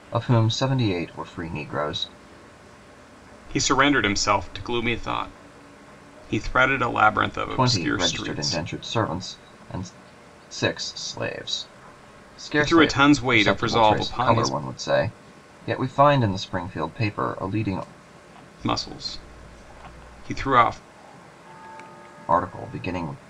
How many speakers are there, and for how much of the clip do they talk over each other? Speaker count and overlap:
two, about 13%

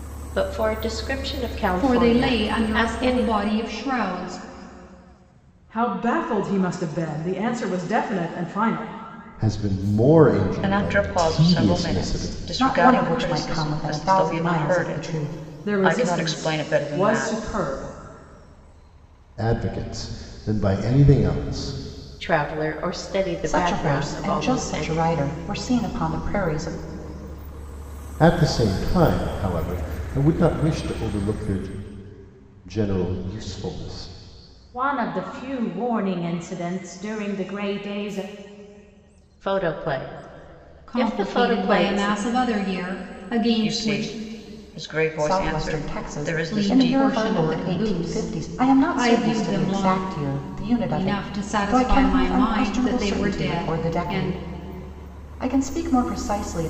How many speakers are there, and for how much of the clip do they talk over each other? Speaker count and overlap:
six, about 35%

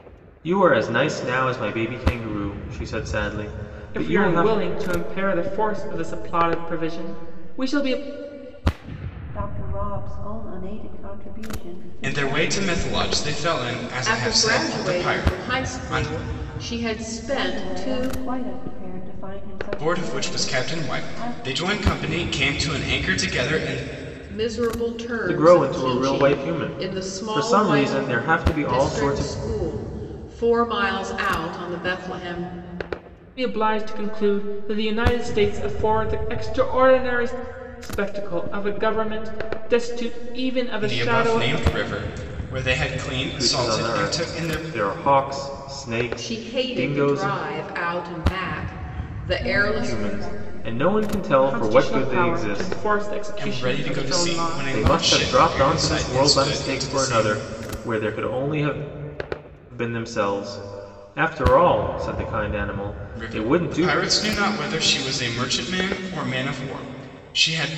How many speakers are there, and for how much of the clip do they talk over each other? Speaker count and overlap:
five, about 33%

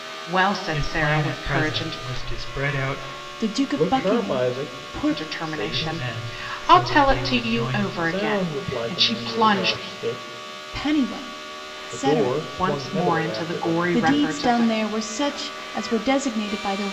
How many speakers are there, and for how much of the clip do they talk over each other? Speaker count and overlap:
four, about 60%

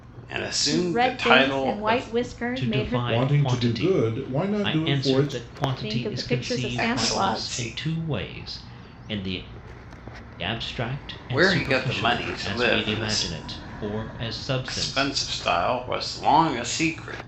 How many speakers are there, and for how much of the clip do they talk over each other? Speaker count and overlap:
four, about 53%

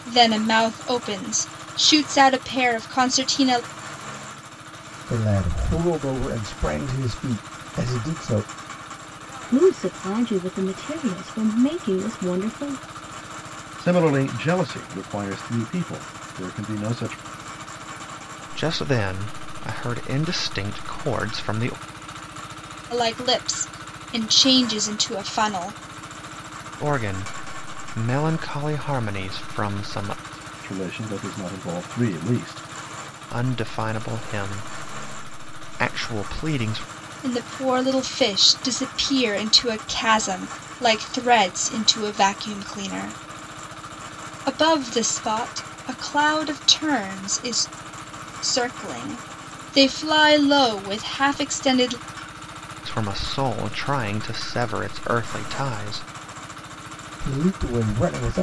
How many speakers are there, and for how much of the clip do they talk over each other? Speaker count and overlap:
five, no overlap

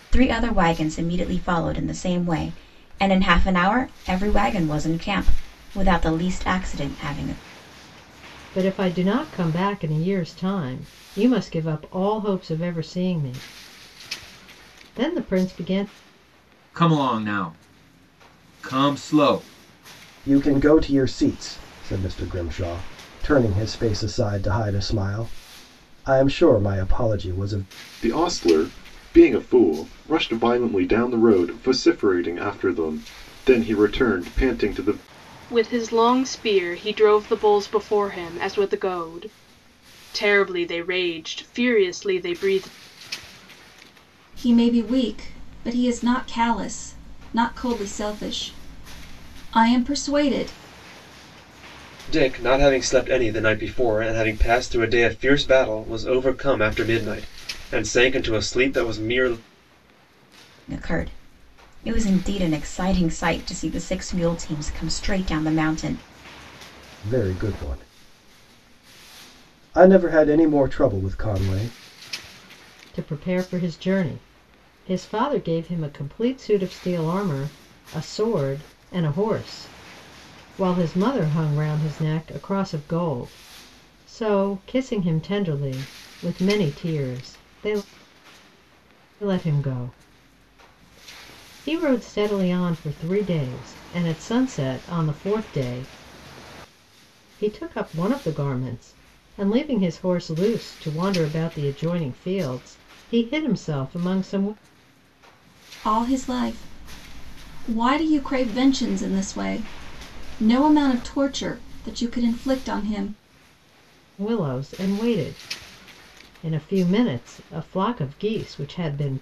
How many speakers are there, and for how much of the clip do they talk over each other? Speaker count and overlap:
eight, no overlap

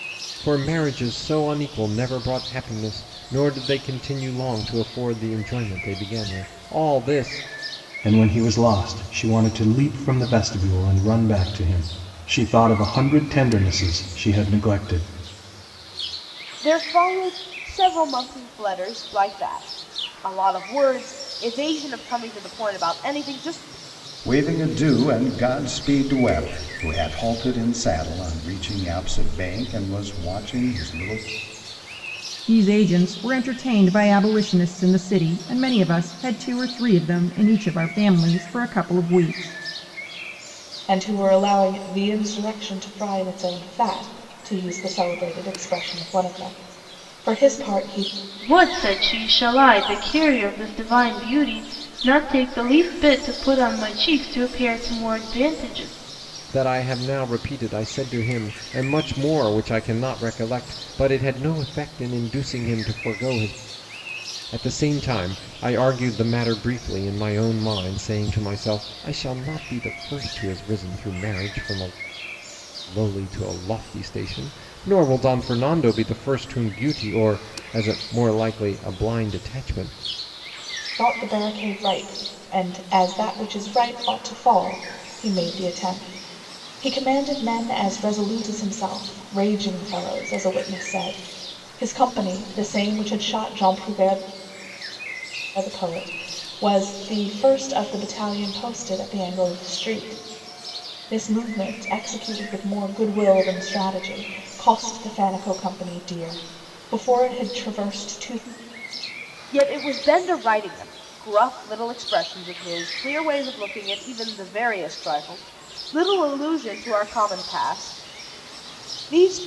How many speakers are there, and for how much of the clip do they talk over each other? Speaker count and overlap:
seven, no overlap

